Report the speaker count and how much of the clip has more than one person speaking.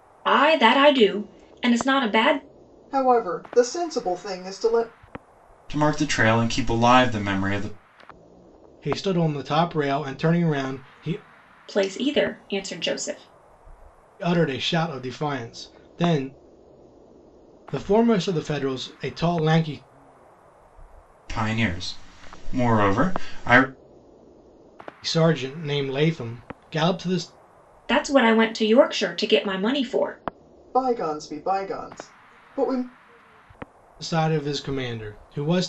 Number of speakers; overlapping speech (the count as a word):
four, no overlap